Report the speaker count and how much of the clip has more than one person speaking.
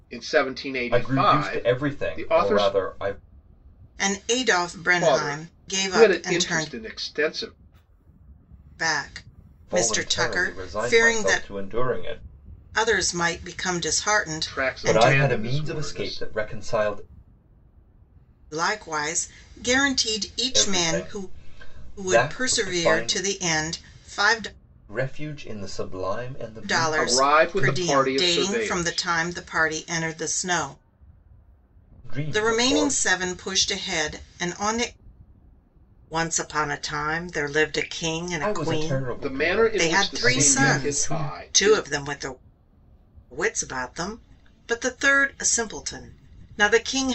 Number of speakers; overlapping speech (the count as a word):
three, about 34%